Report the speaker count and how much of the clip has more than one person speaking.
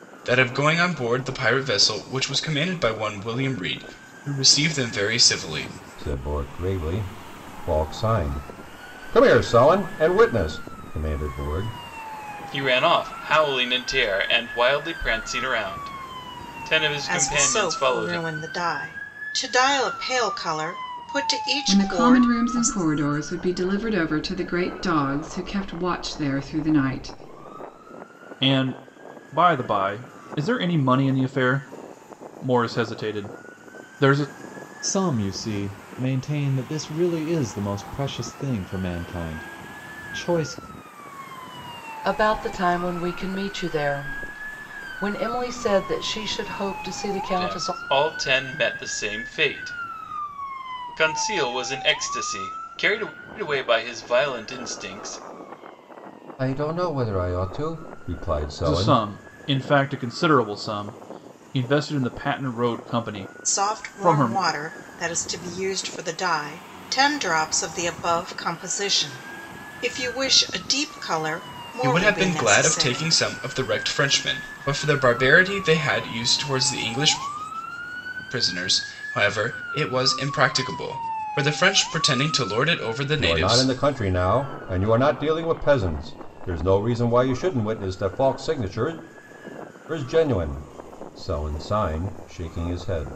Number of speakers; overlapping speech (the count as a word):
eight, about 6%